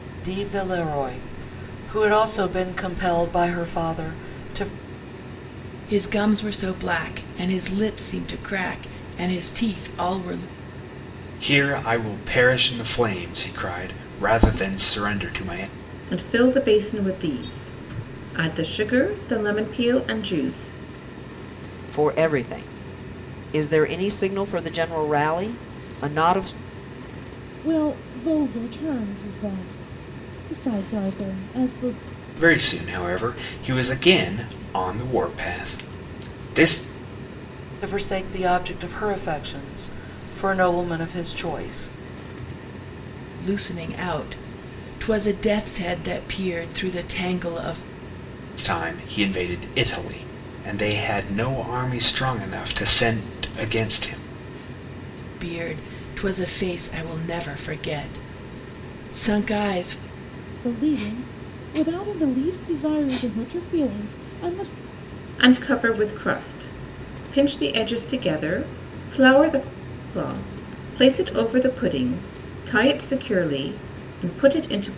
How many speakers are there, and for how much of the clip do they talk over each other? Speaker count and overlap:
6, no overlap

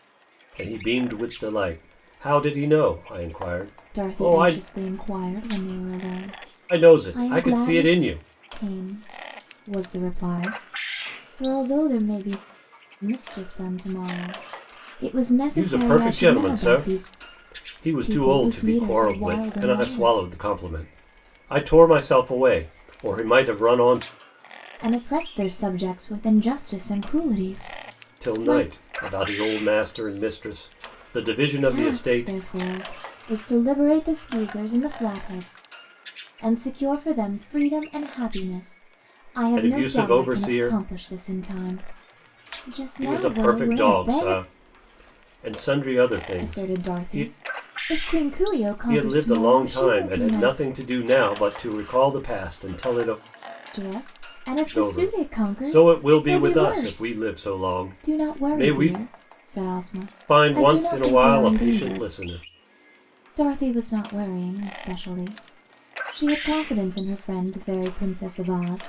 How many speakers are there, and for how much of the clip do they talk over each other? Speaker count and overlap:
2, about 26%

